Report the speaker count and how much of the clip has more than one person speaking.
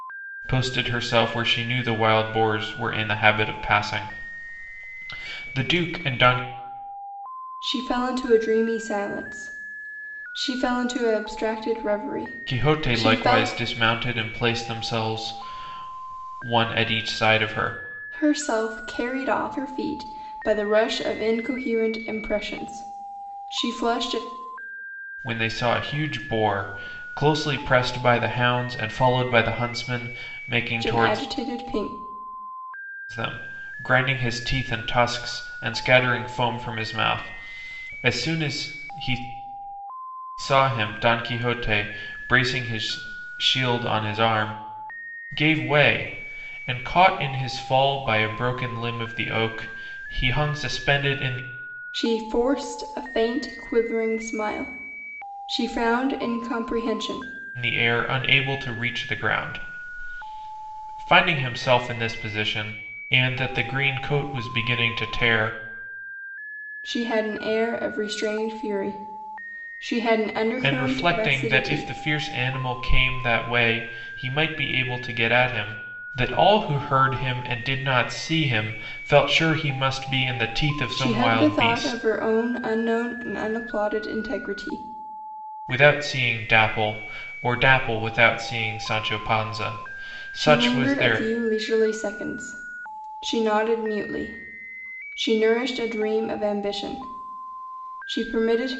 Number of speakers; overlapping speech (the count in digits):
2, about 5%